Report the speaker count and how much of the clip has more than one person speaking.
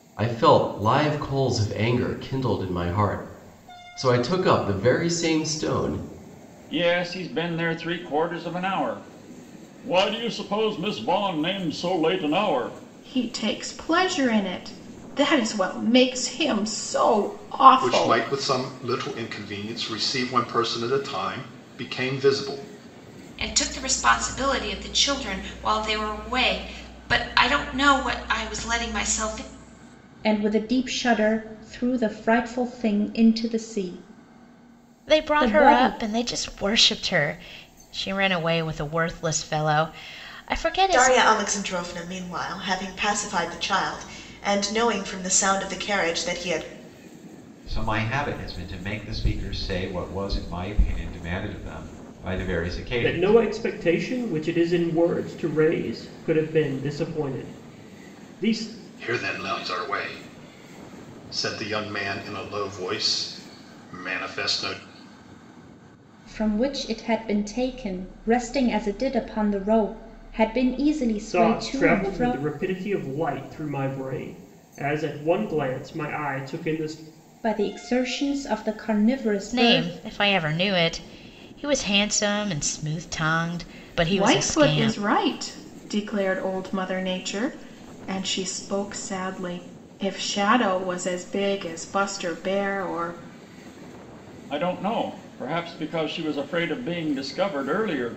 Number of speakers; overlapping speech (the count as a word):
ten, about 5%